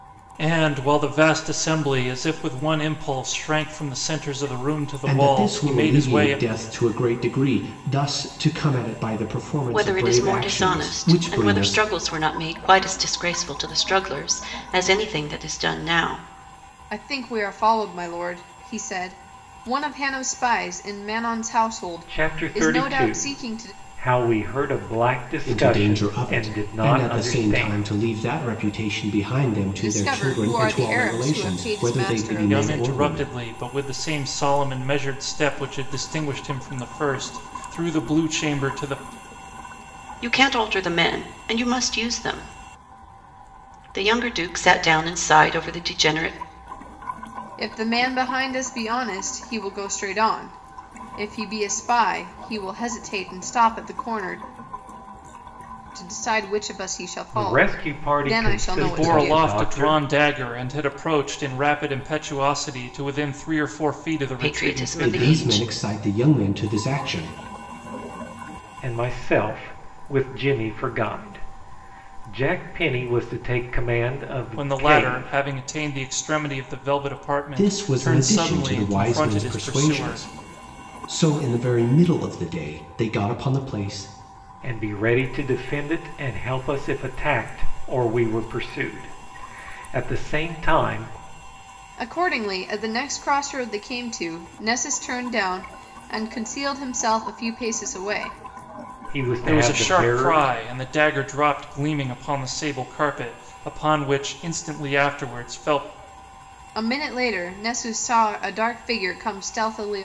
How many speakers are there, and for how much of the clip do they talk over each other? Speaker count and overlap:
5, about 18%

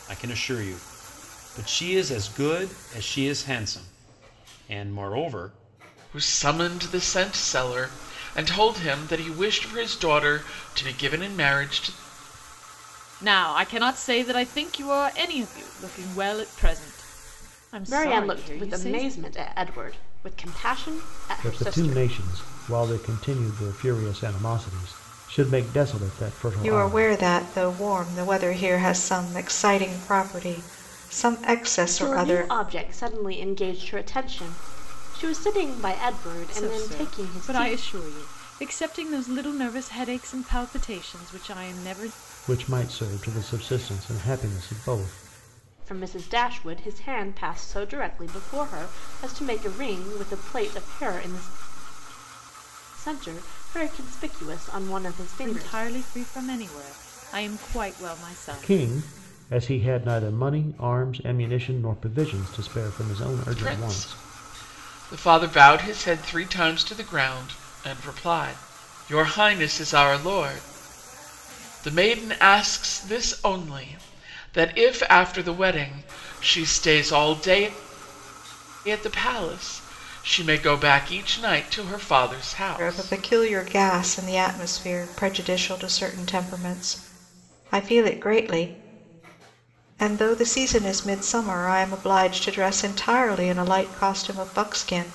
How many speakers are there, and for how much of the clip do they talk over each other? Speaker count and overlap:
6, about 7%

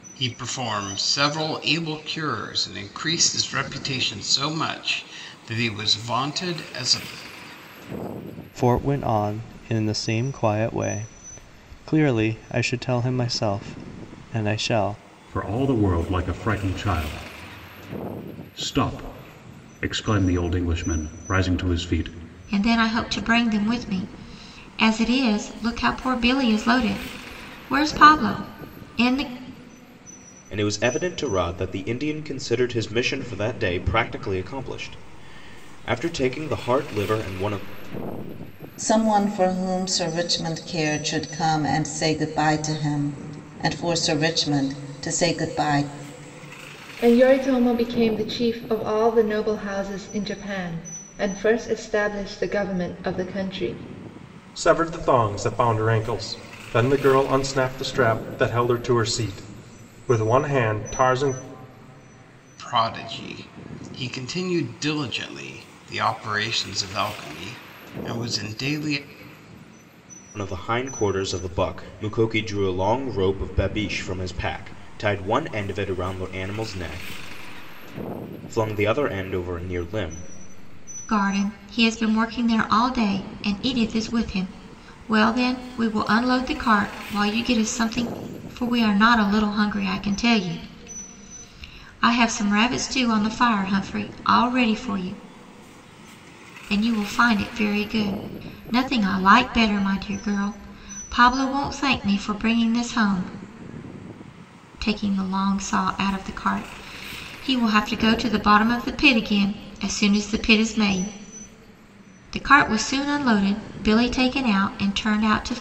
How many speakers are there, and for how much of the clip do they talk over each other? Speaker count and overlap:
8, no overlap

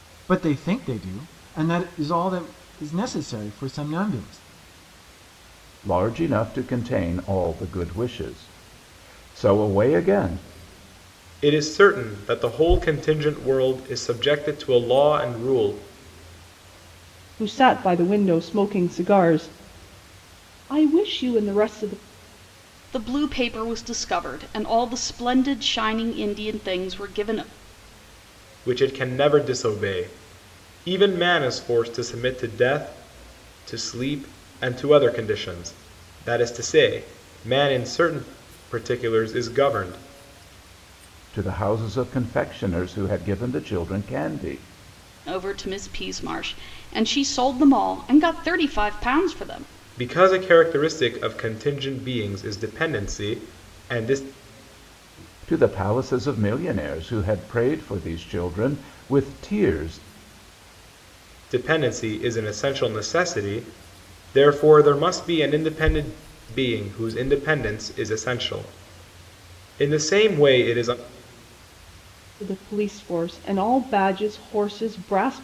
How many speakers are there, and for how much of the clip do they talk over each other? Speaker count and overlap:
5, no overlap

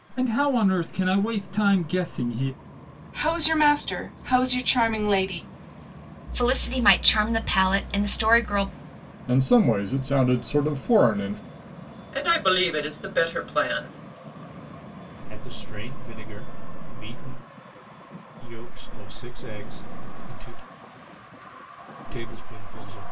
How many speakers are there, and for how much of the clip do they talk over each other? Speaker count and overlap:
6, no overlap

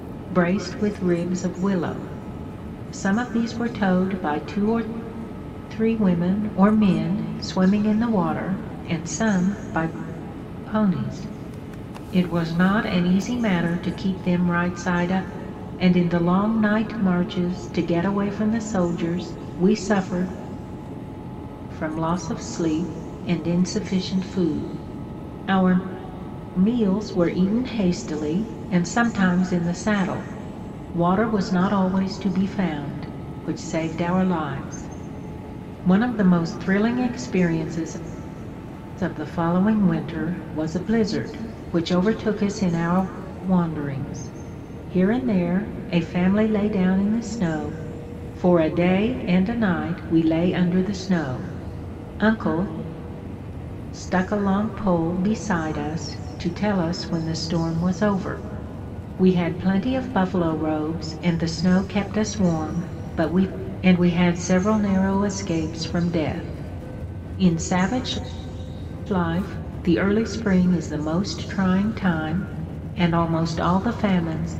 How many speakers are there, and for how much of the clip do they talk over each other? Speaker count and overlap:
1, no overlap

